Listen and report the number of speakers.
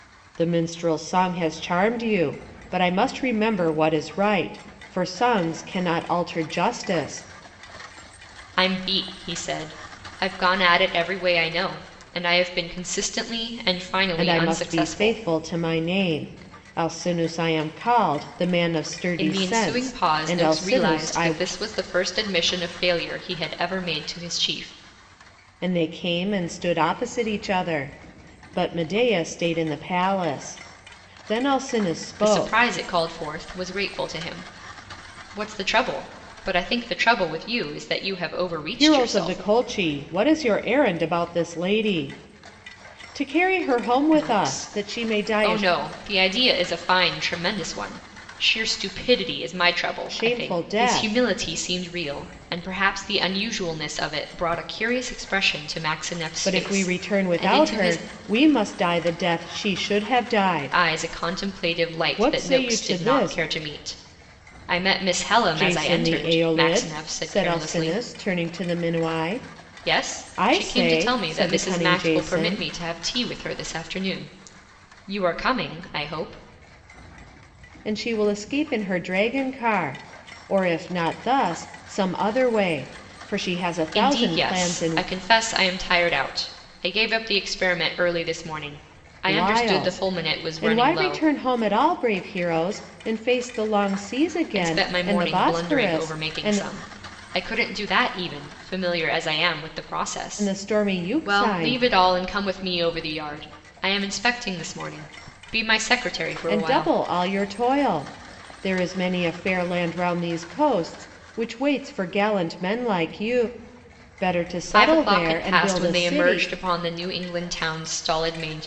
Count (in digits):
2